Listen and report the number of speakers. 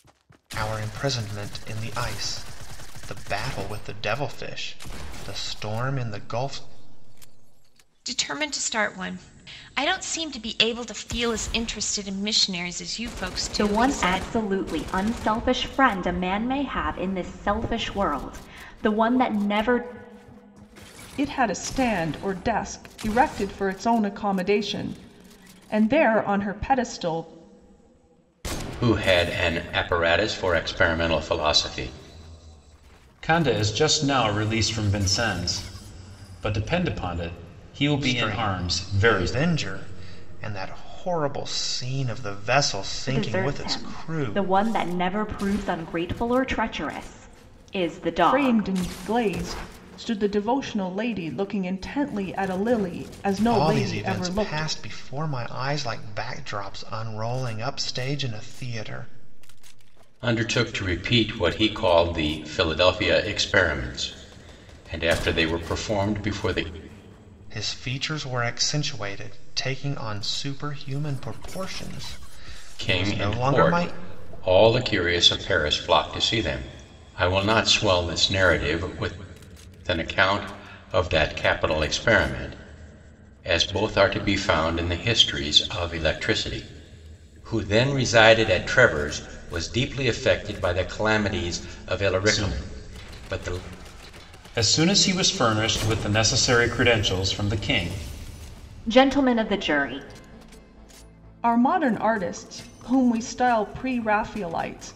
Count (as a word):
six